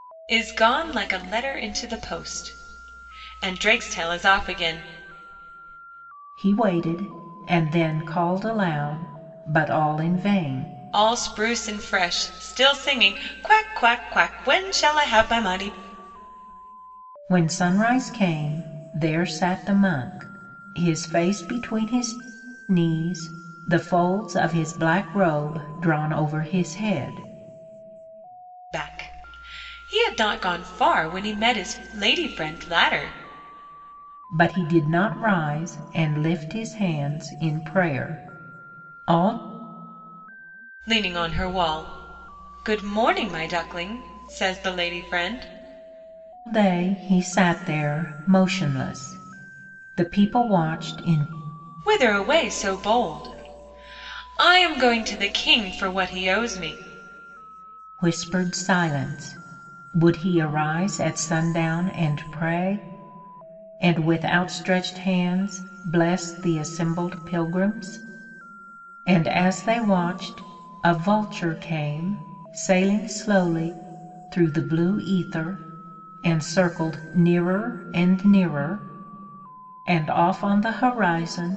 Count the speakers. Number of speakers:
2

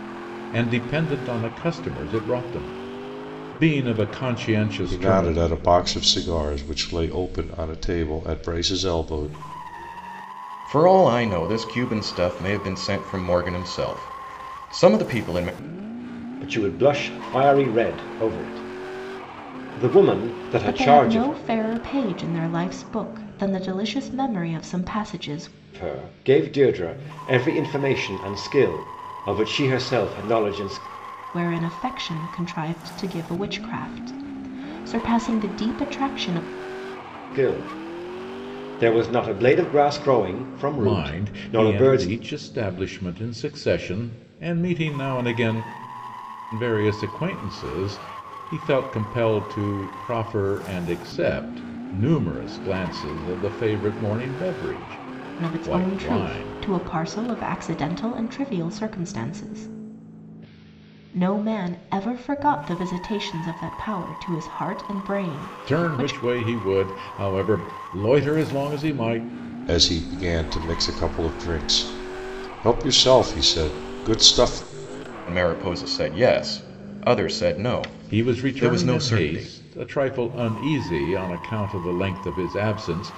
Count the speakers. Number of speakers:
5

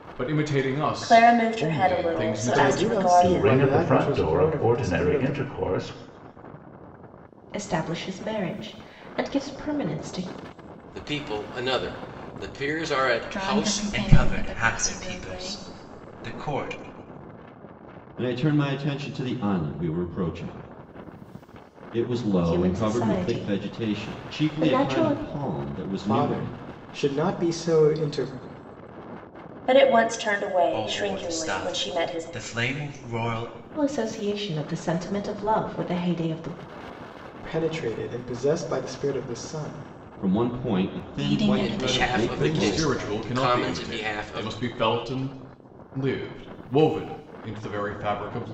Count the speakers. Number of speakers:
9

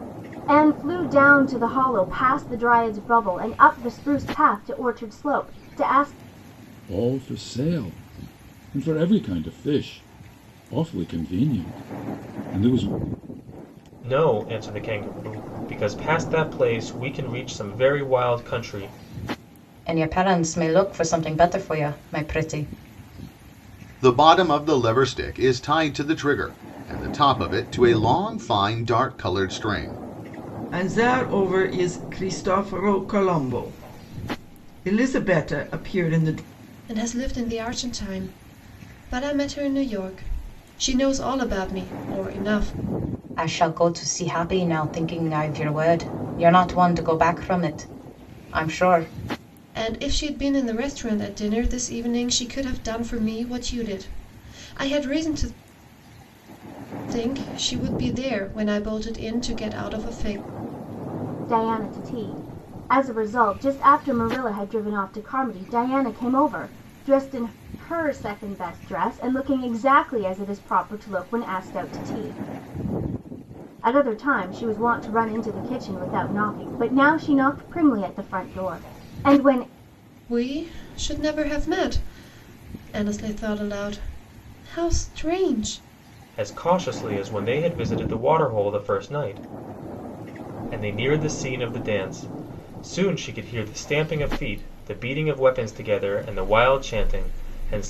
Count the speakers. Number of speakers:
7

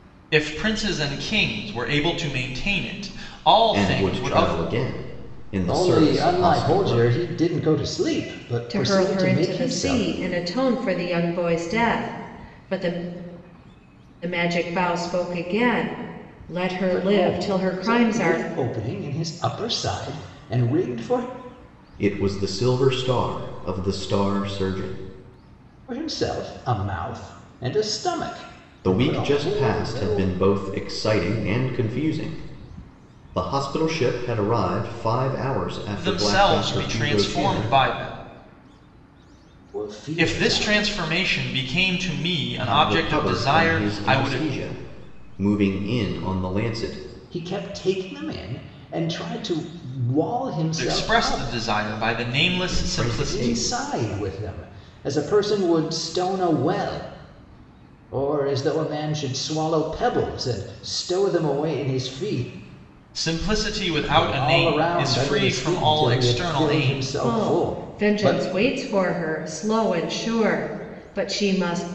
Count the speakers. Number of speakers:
4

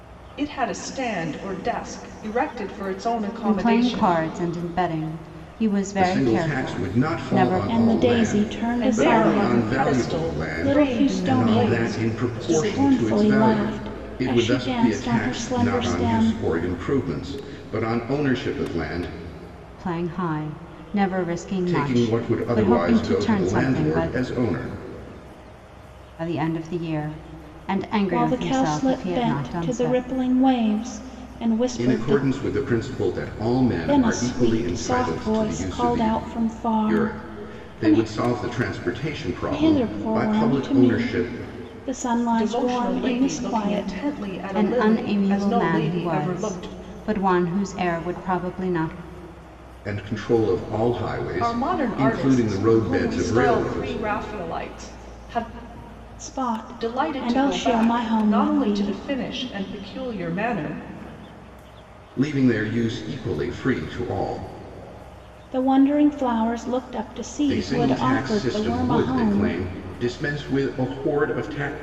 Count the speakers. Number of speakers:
4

